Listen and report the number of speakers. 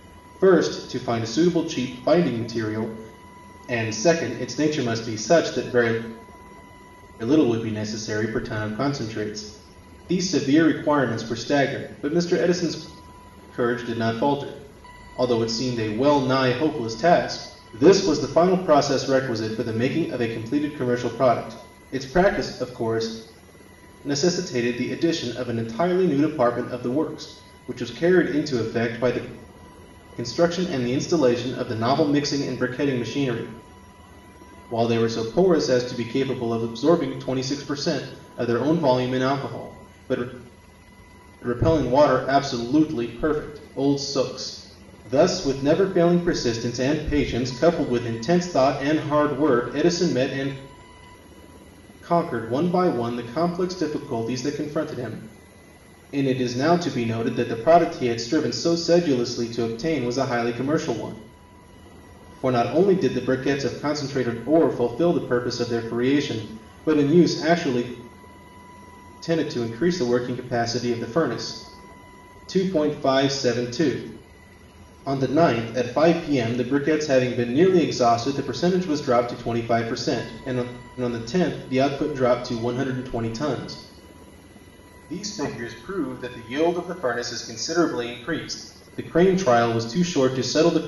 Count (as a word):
one